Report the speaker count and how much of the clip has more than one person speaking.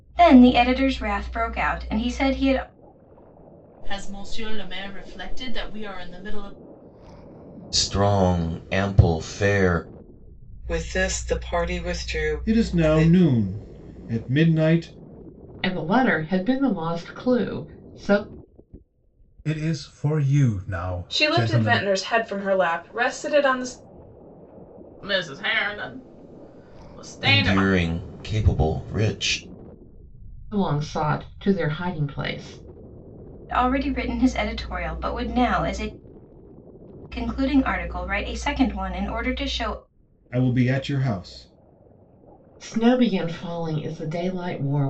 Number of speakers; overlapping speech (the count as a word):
nine, about 4%